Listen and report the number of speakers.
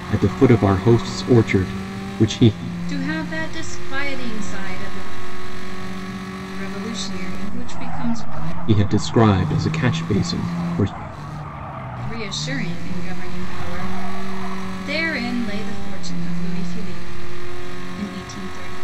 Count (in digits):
2